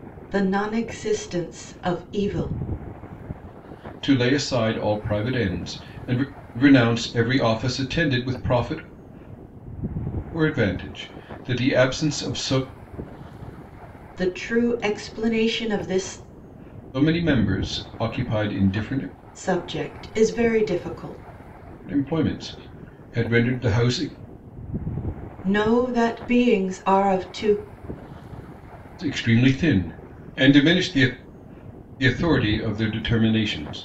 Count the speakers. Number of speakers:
2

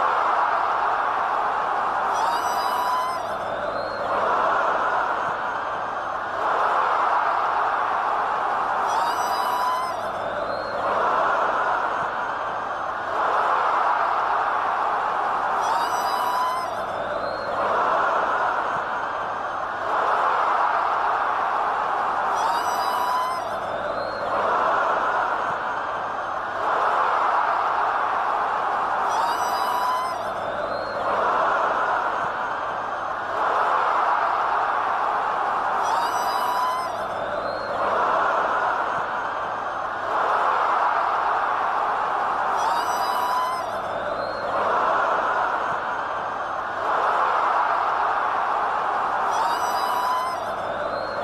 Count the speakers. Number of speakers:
0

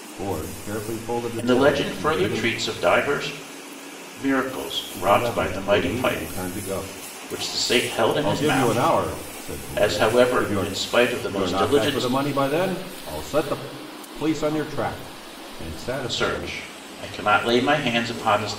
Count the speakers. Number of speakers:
2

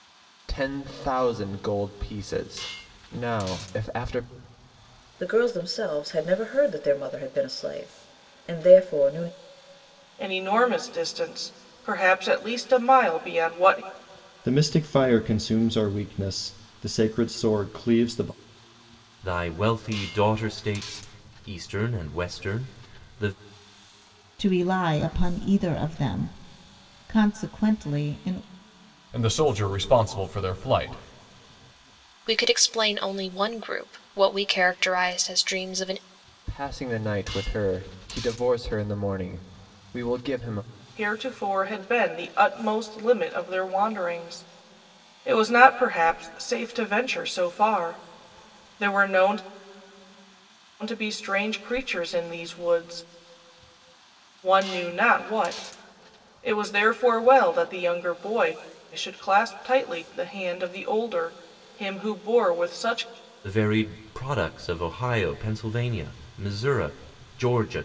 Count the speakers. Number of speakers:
8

